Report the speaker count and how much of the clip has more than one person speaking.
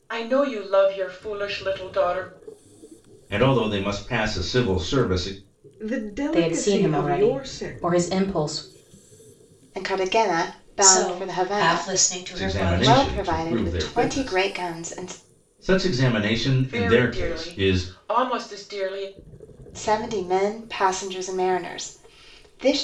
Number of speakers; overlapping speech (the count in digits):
6, about 26%